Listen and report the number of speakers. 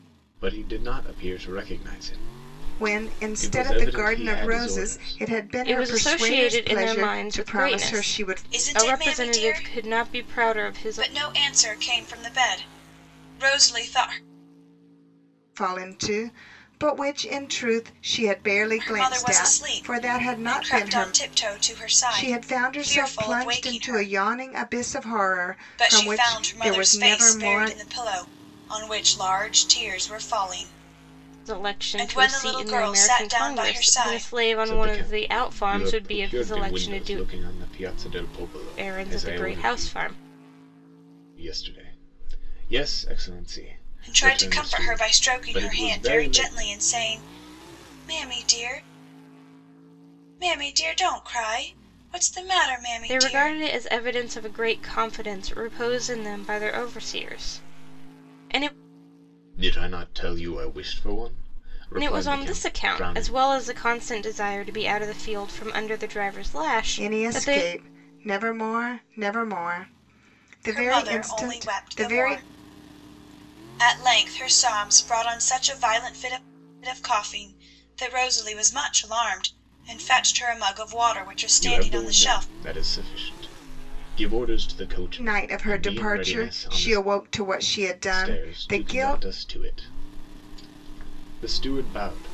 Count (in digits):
4